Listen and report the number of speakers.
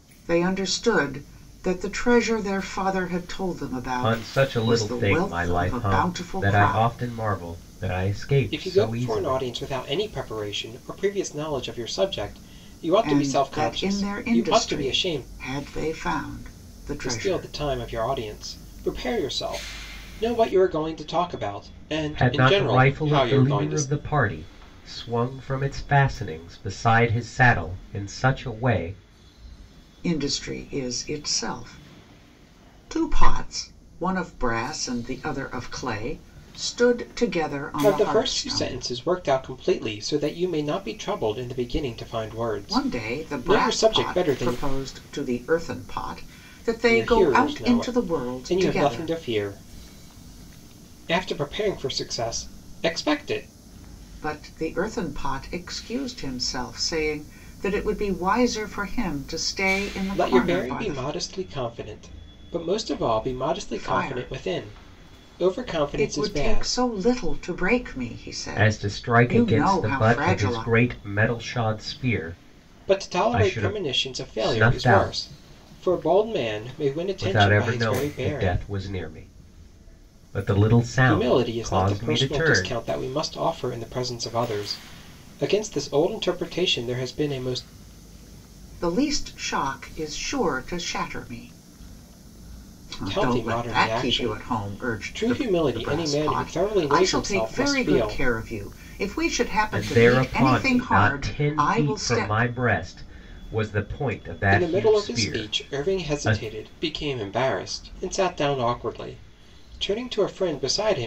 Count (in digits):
3